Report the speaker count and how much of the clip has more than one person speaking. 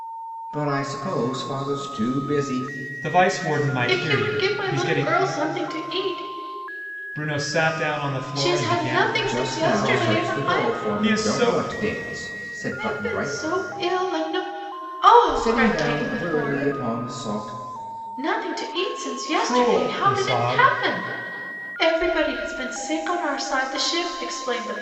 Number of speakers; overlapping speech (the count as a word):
three, about 32%